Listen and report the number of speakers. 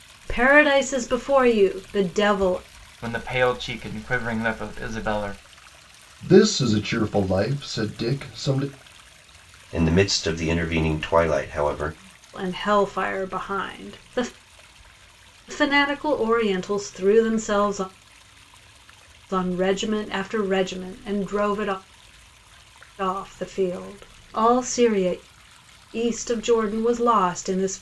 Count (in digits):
4